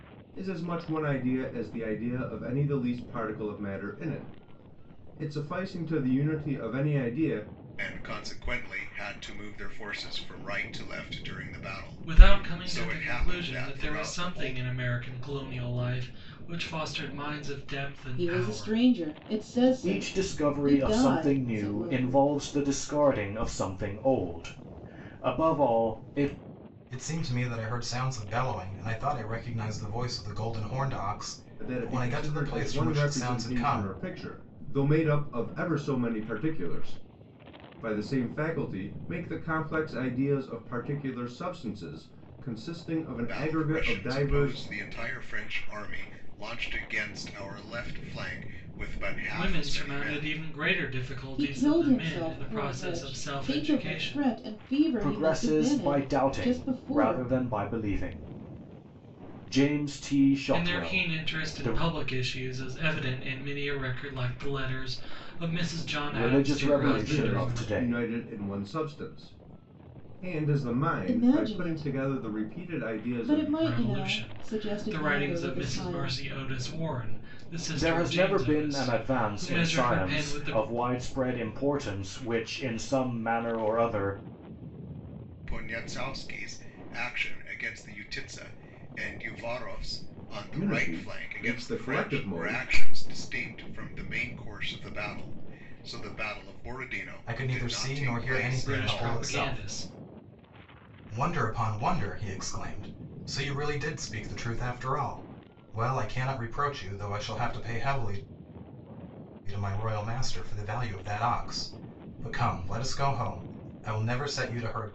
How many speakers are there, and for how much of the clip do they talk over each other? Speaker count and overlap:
6, about 28%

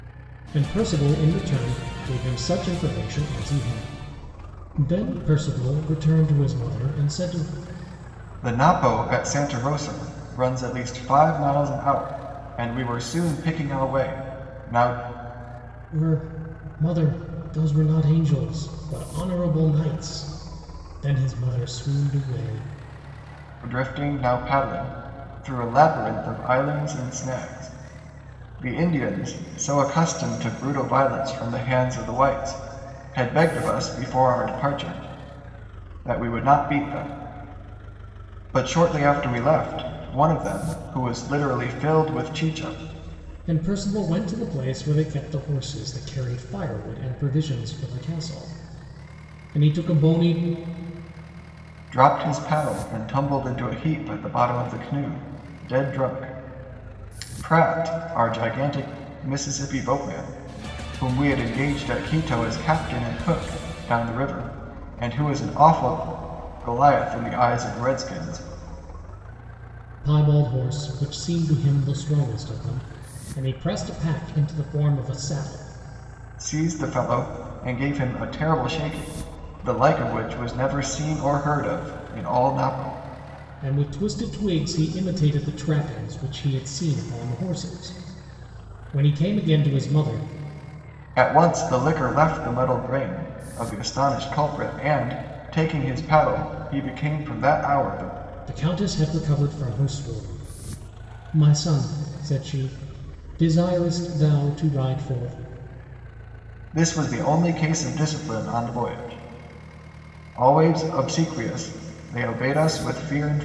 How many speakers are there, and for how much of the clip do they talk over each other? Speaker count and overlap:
2, no overlap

